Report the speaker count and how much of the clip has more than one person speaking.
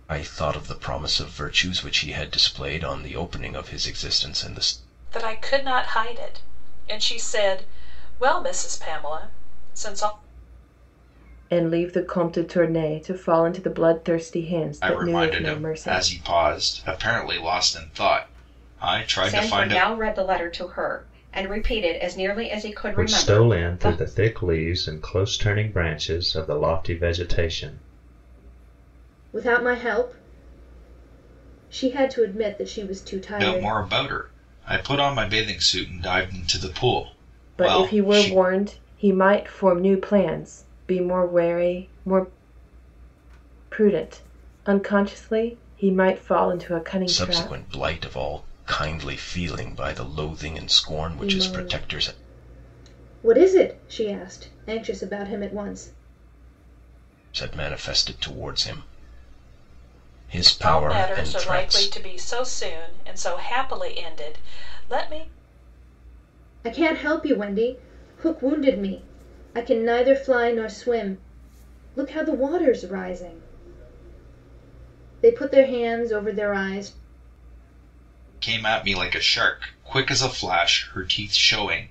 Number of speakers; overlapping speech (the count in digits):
7, about 9%